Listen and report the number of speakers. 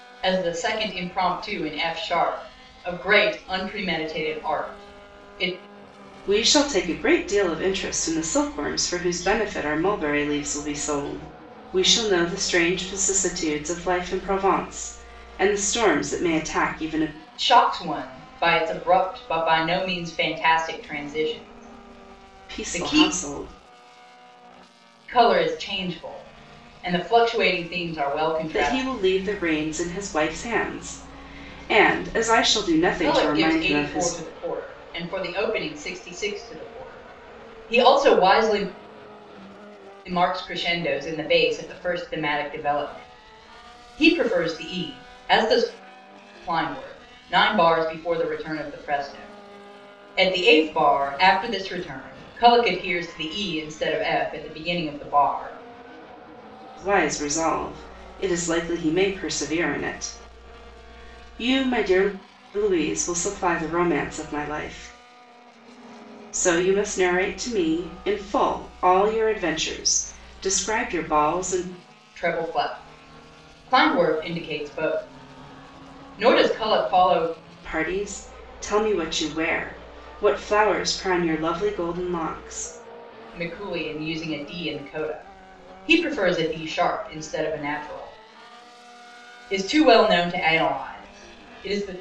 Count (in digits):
2